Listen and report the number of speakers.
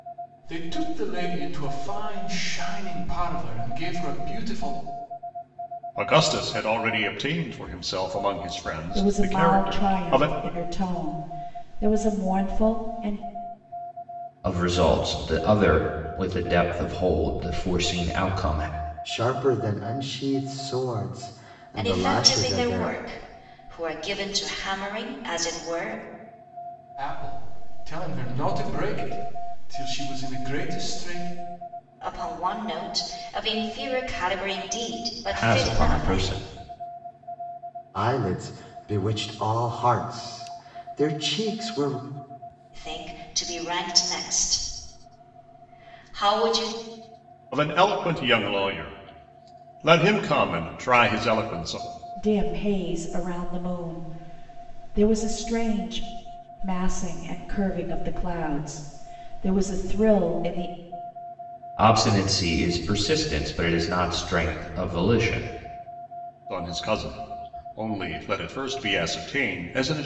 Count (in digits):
6